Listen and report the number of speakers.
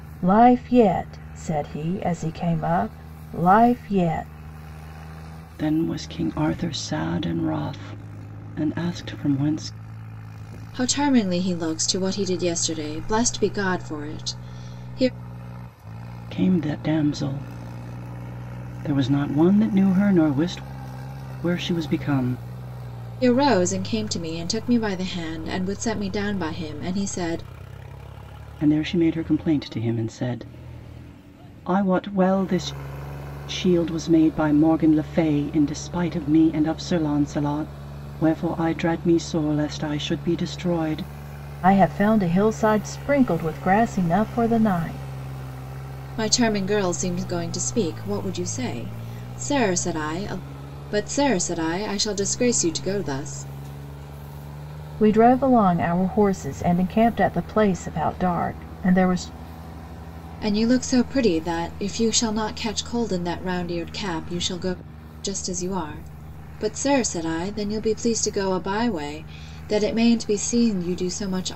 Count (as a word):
three